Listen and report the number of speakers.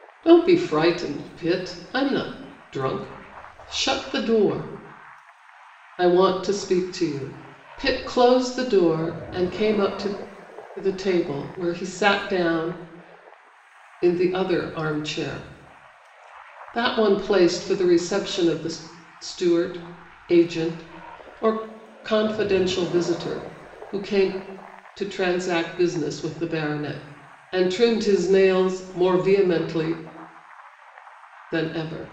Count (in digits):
1